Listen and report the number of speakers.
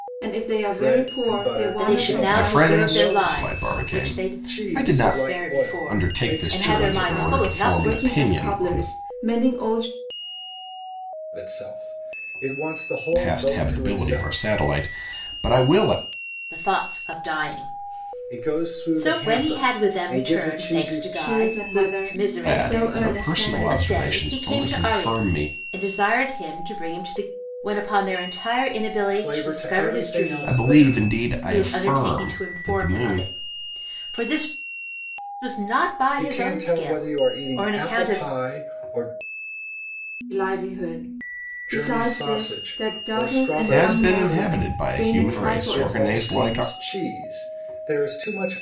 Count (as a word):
four